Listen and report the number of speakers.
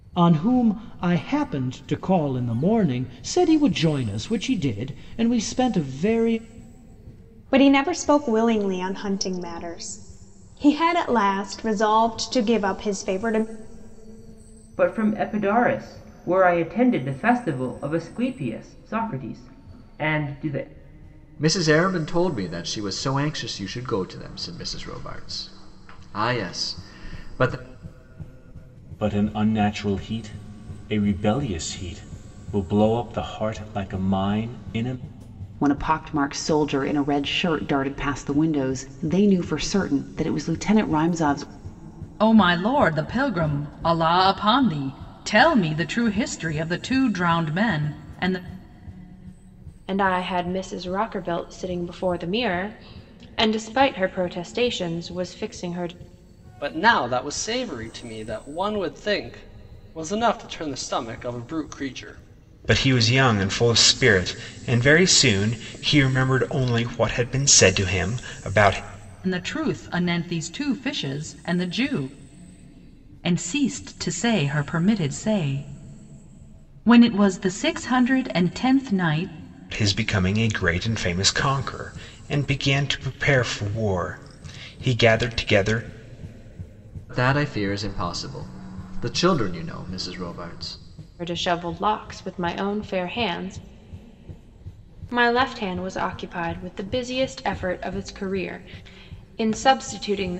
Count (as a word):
ten